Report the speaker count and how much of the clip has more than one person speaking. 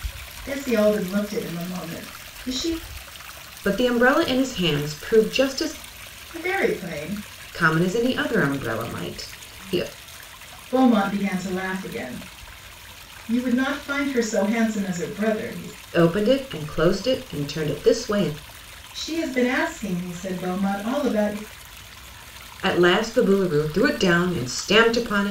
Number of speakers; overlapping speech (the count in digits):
2, no overlap